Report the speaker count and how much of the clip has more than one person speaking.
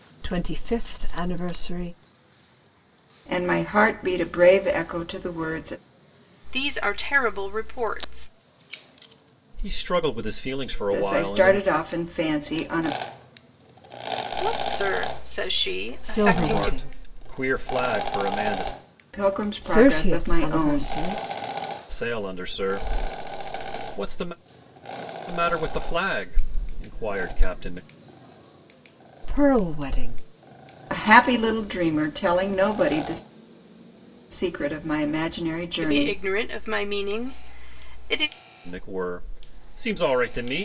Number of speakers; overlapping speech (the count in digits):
4, about 8%